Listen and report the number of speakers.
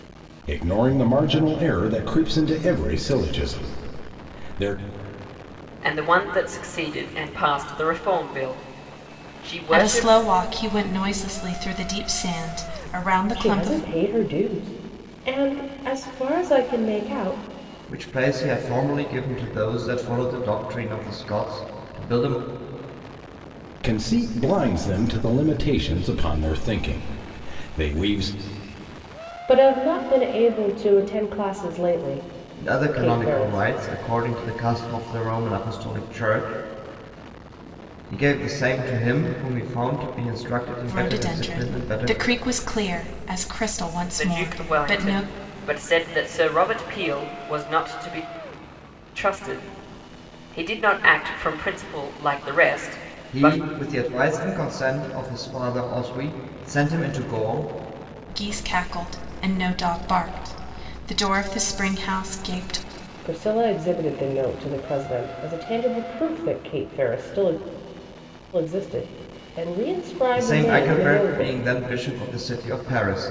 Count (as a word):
five